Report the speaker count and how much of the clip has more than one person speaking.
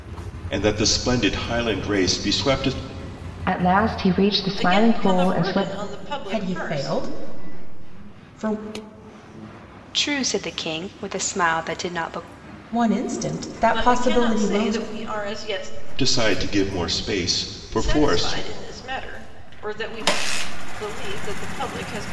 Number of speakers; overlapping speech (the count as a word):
five, about 18%